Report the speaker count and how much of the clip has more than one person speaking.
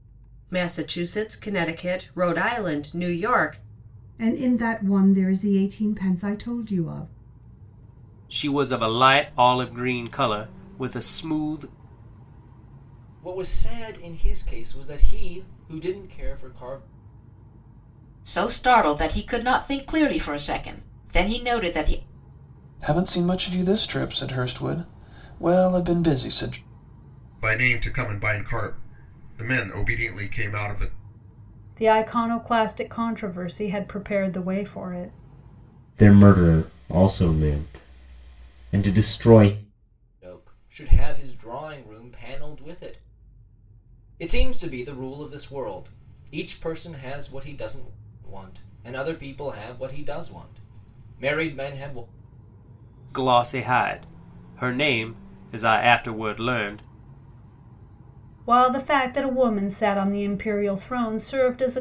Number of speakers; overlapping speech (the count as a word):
nine, no overlap